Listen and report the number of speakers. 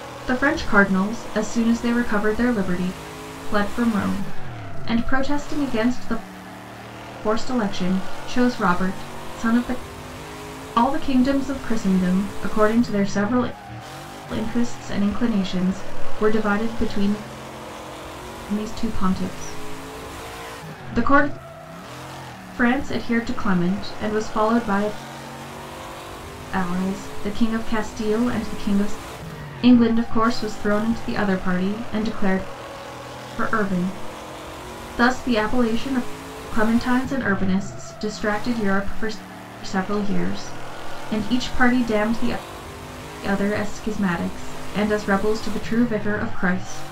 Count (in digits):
1